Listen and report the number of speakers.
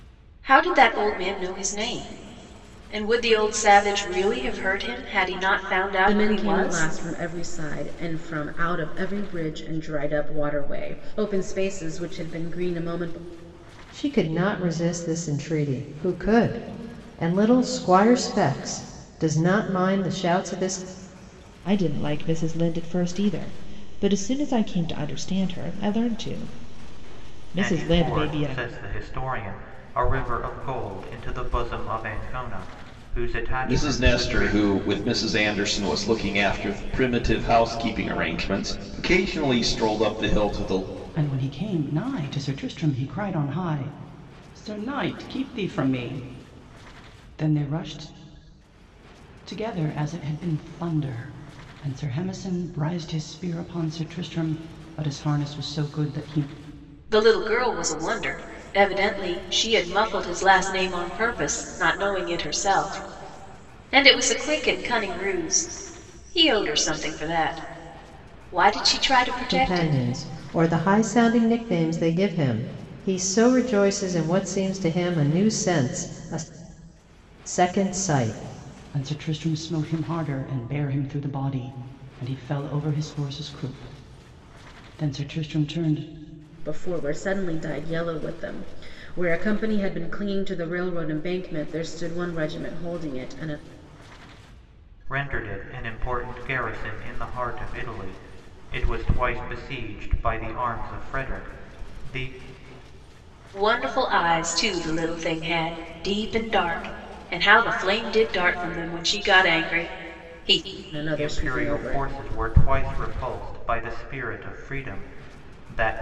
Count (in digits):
7